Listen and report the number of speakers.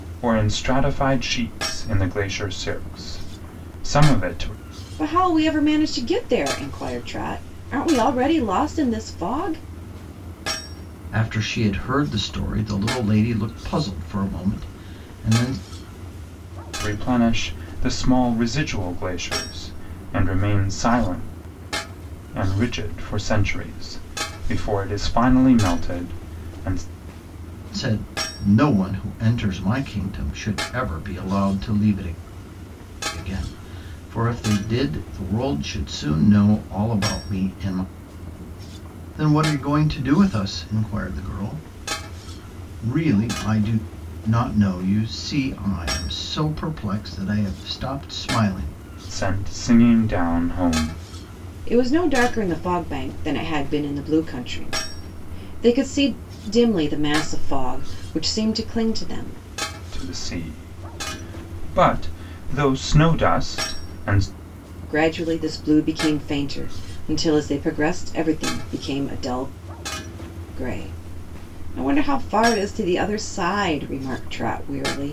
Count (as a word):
three